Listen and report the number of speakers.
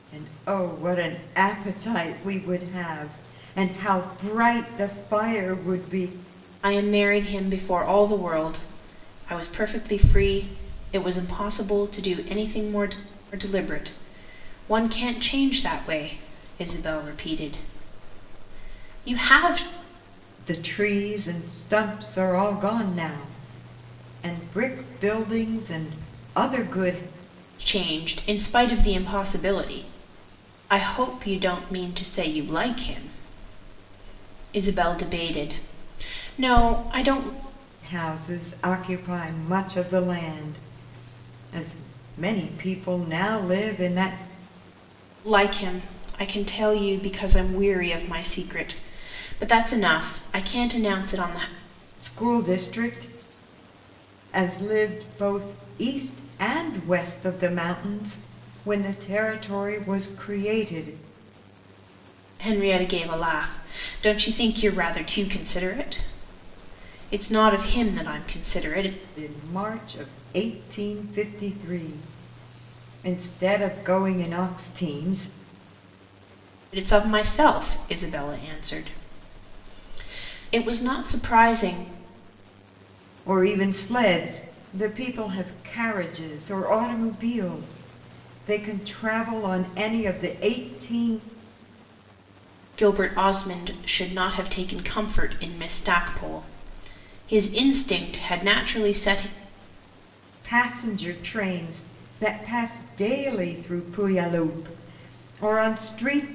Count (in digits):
2